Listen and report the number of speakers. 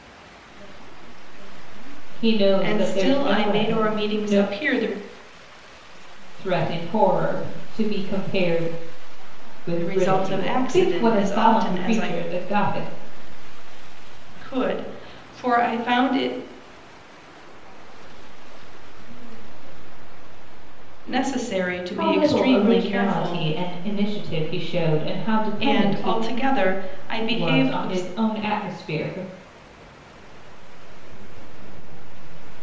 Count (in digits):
3